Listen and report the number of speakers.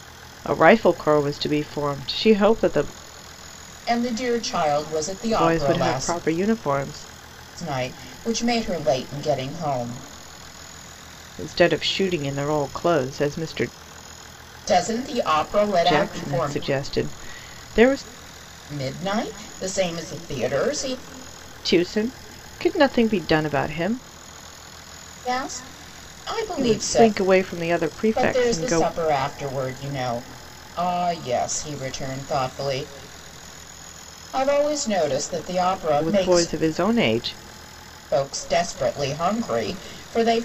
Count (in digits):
2